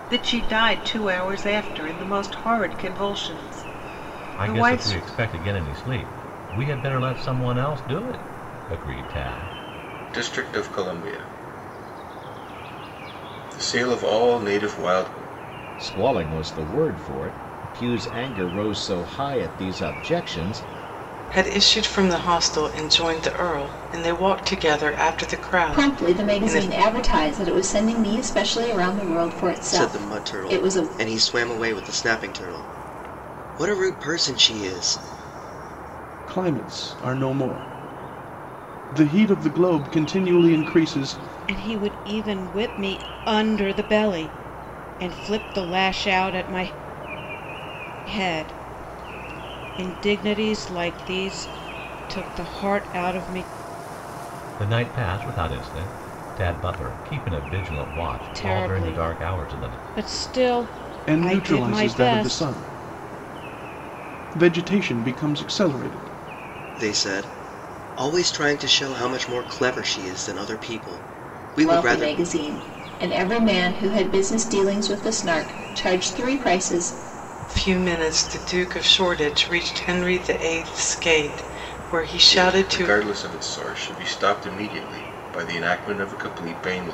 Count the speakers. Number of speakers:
nine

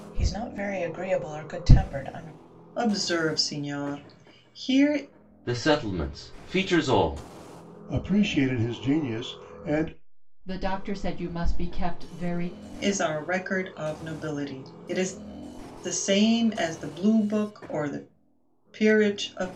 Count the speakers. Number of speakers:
five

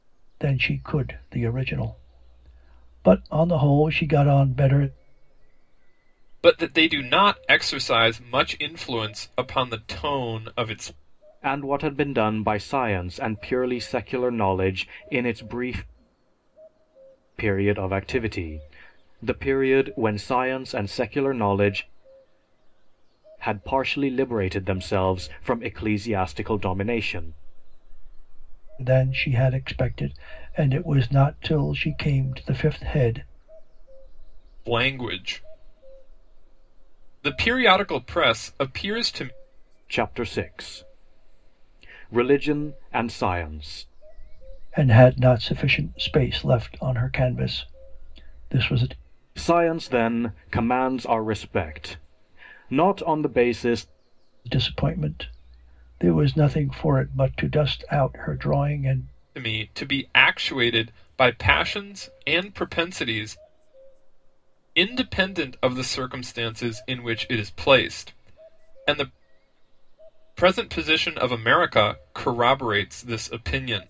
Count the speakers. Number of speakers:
three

